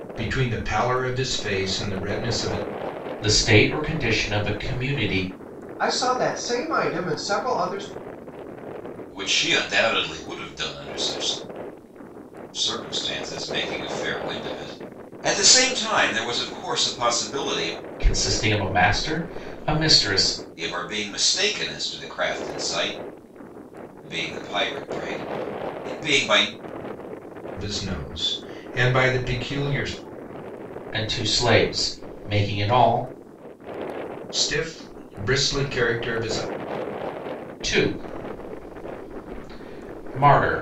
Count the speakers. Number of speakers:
4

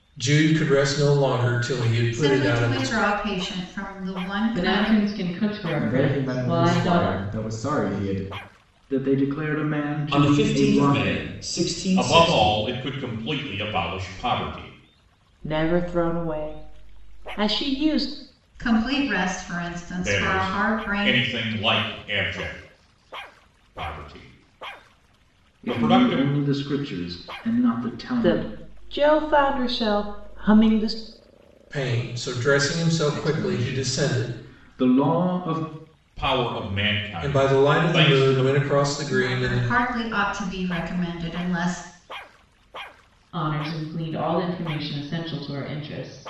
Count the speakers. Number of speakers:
8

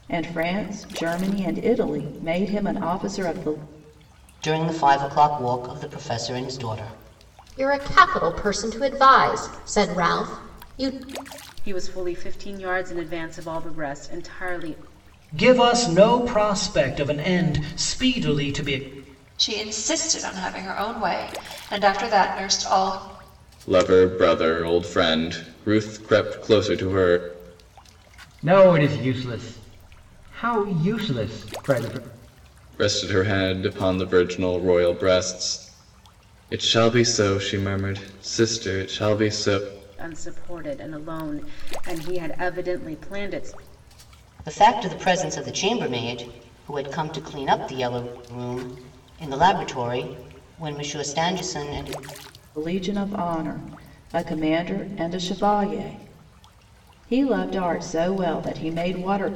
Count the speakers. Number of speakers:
8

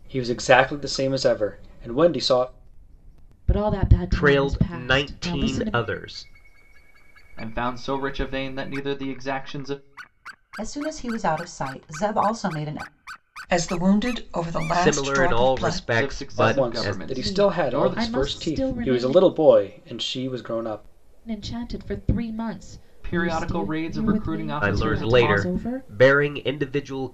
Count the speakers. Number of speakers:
6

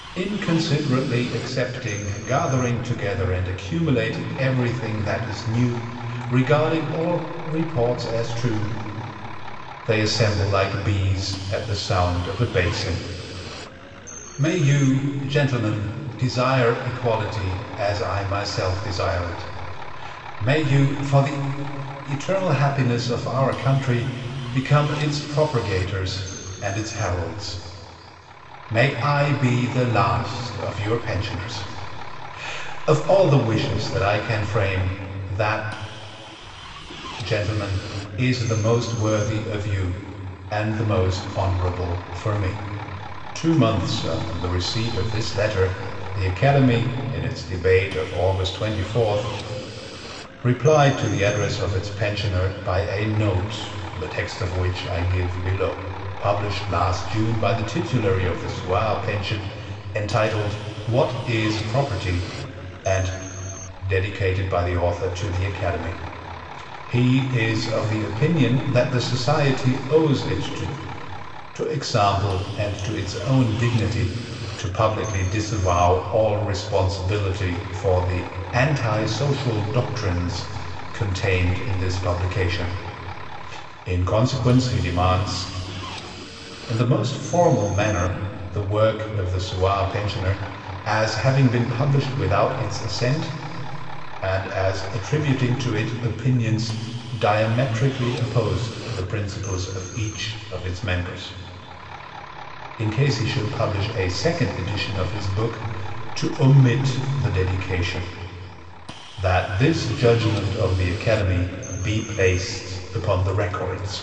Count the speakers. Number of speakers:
1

